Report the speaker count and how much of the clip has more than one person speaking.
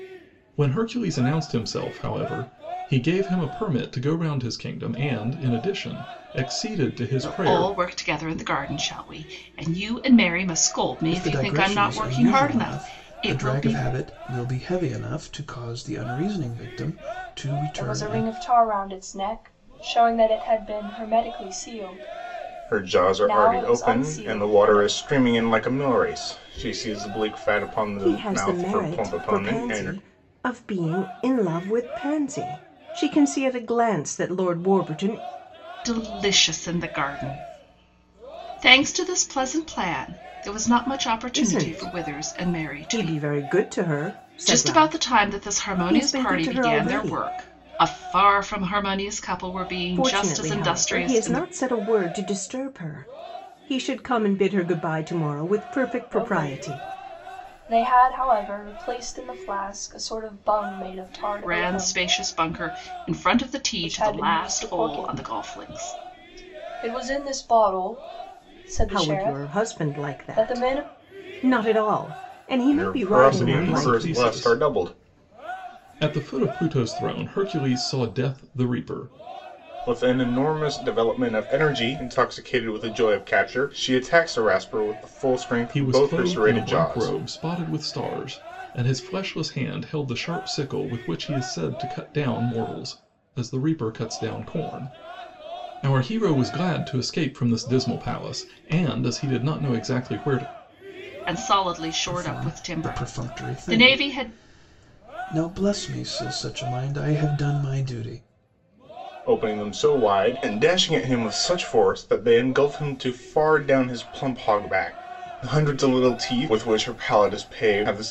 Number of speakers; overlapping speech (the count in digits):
6, about 22%